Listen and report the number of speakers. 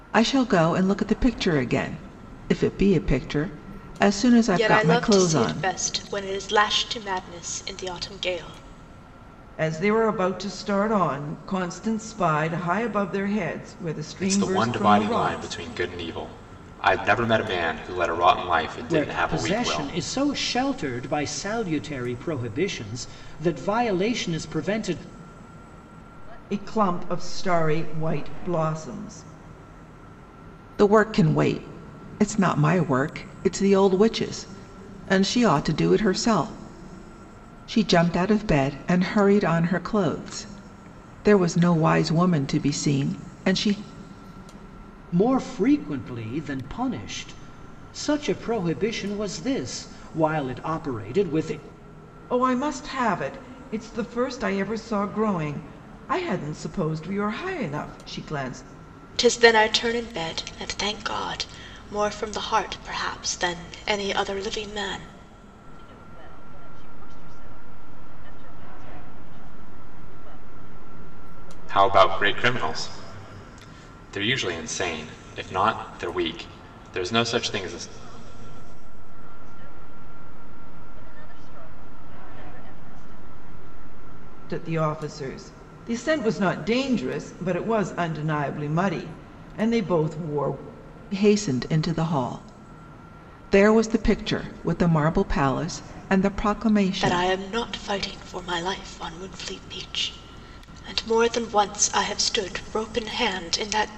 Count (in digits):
6